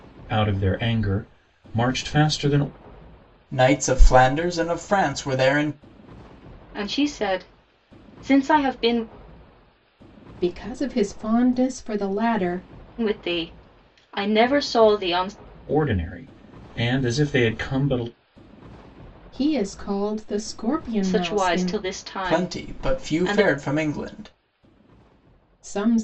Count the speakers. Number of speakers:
4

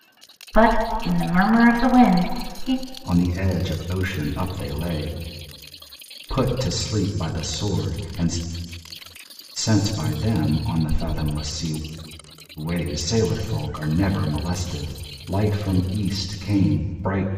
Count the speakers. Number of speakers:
2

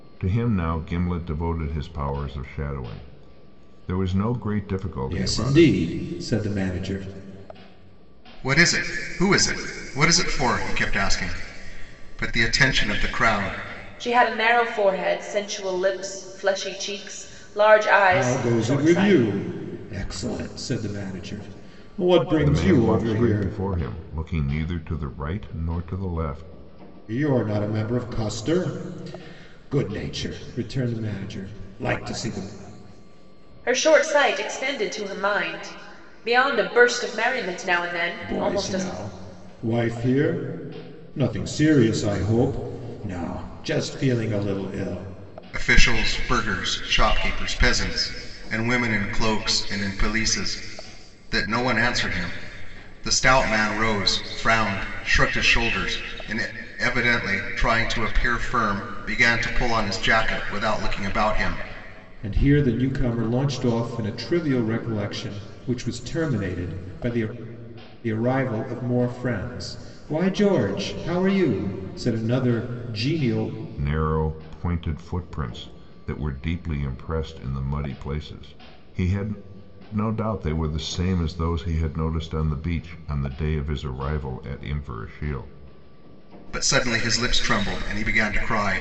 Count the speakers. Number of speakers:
4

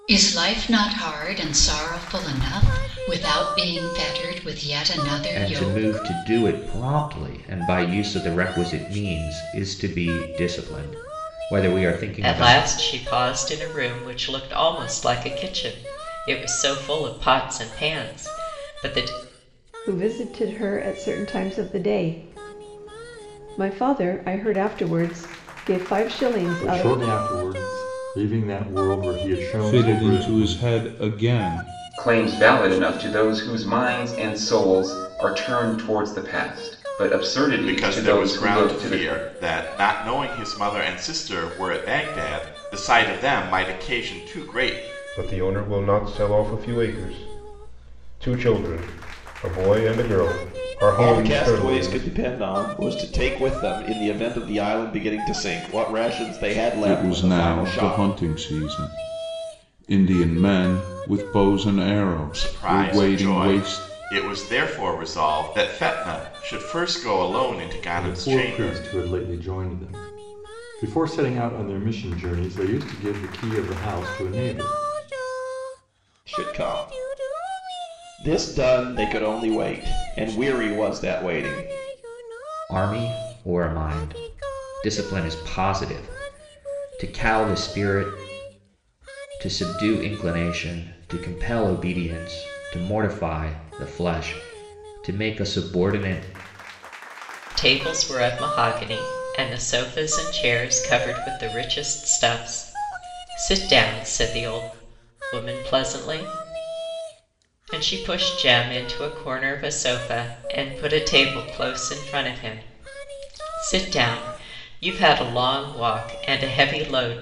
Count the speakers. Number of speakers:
10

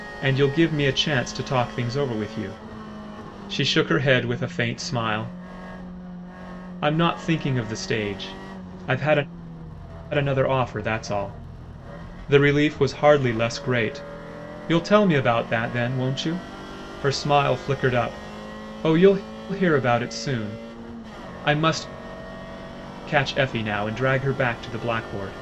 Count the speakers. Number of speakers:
1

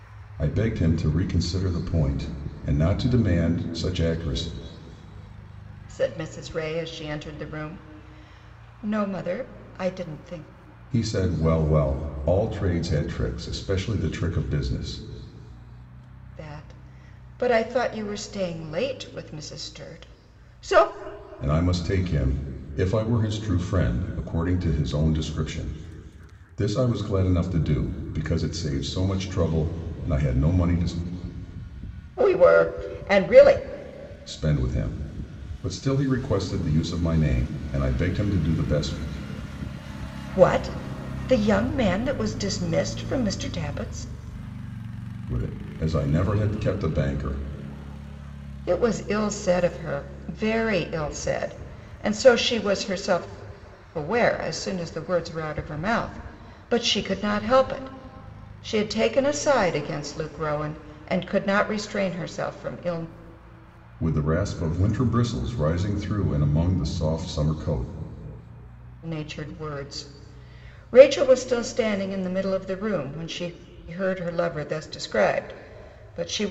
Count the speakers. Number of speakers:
2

